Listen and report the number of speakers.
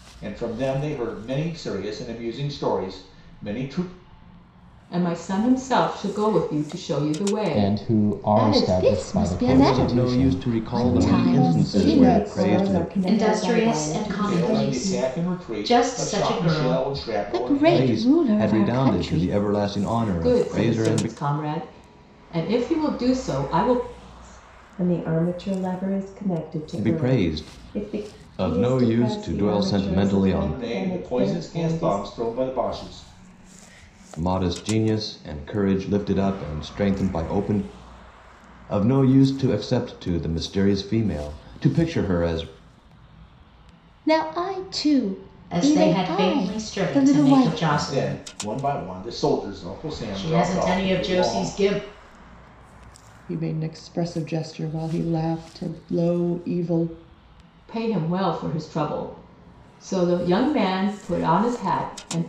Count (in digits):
8